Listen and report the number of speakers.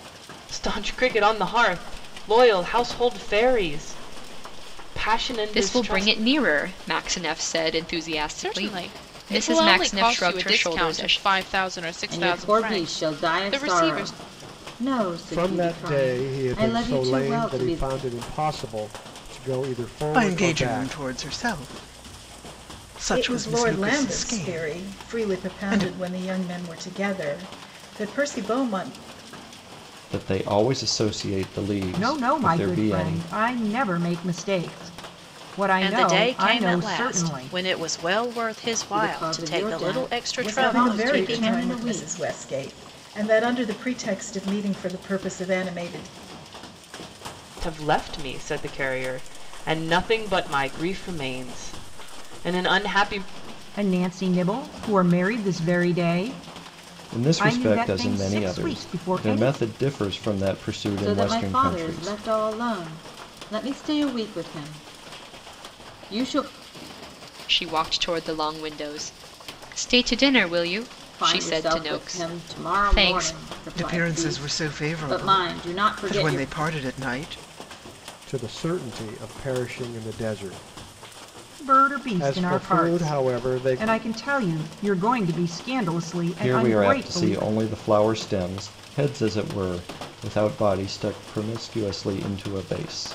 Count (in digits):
10